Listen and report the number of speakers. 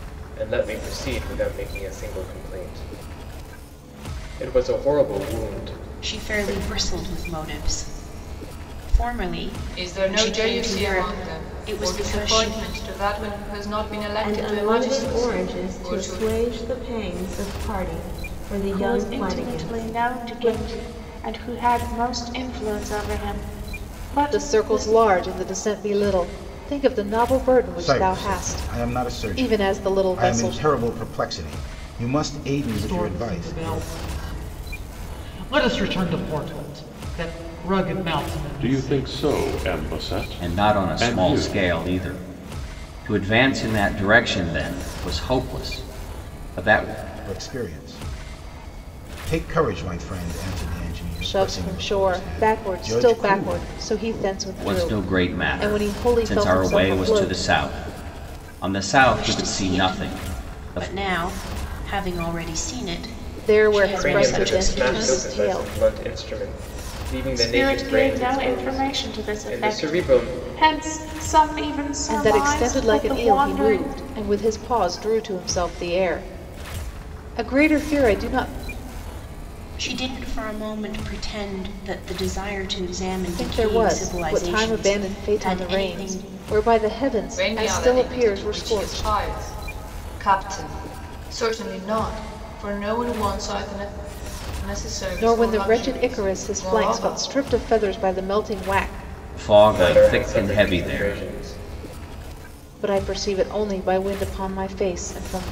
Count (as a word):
ten